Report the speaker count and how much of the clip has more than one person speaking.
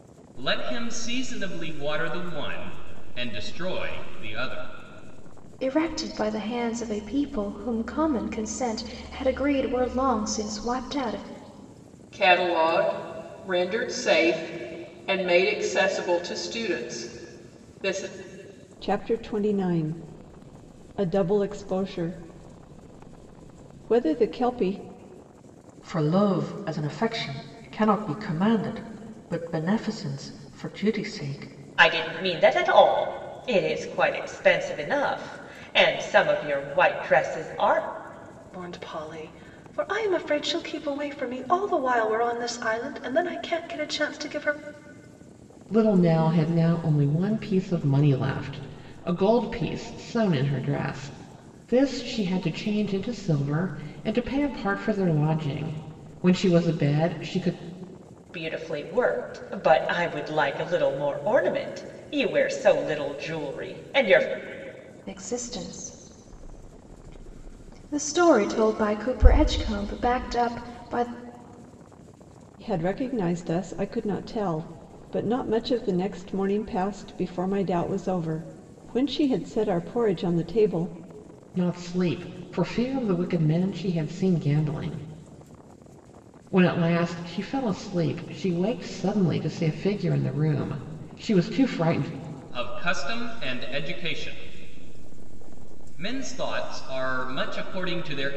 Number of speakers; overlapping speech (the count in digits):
8, no overlap